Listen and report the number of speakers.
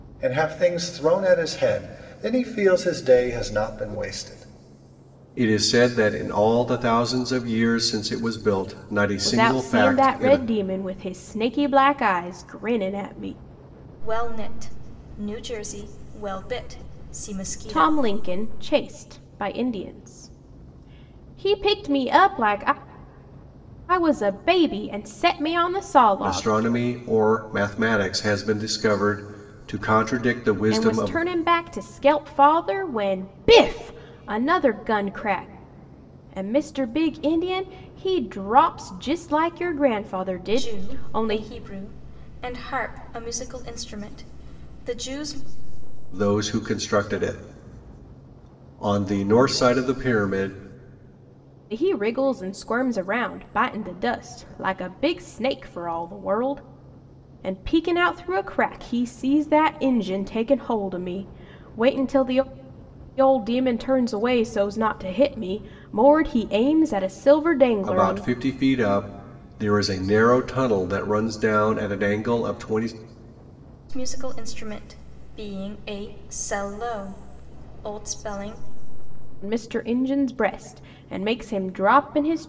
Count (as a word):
four